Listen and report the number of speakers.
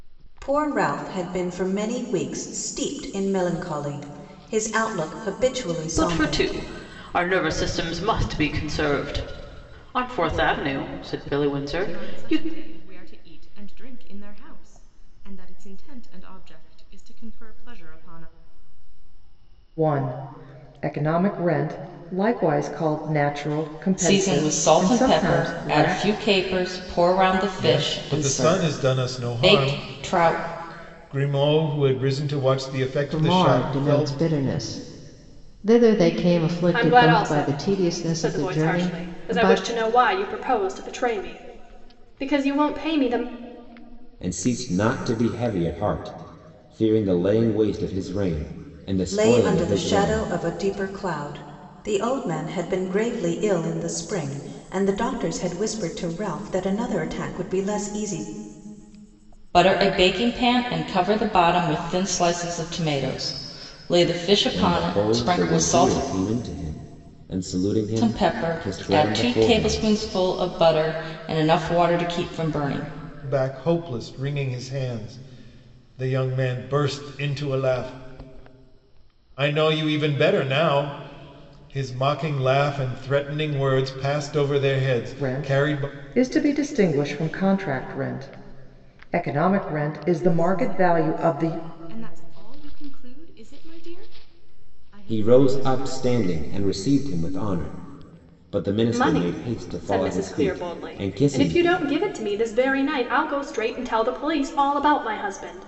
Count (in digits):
9